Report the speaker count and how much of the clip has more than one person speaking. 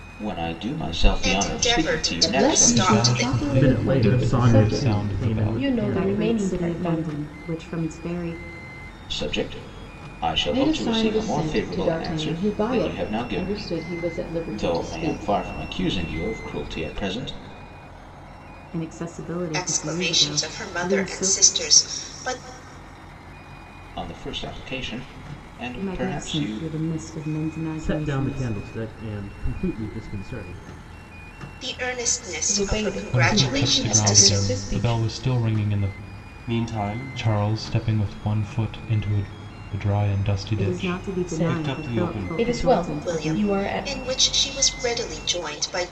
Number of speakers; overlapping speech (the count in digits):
7, about 43%